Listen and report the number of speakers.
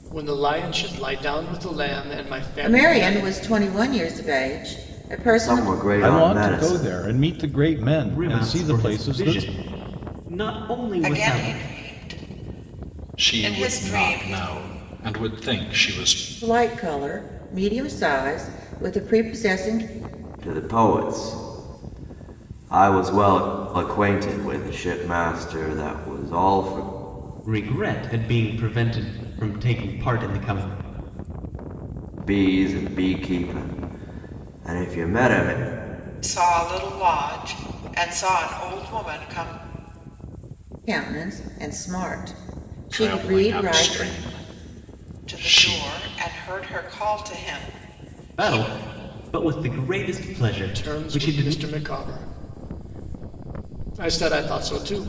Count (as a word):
seven